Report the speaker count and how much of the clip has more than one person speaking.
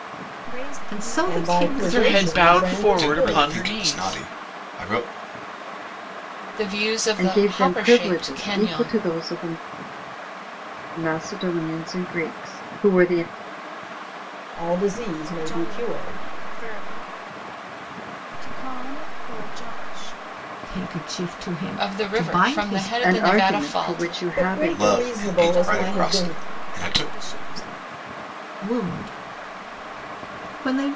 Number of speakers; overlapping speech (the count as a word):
seven, about 37%